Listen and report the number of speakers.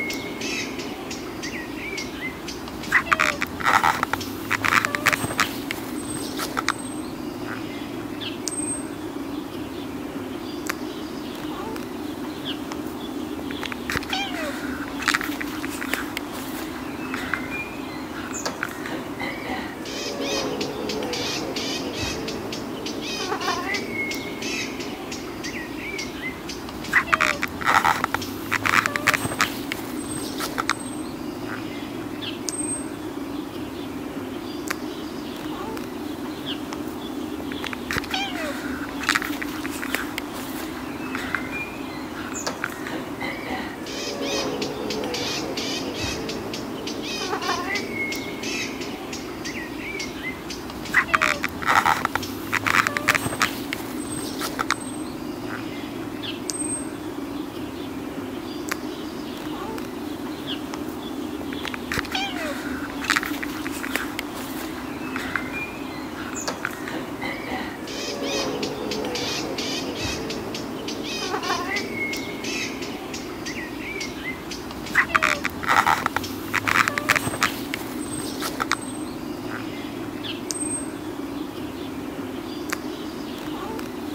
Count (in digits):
0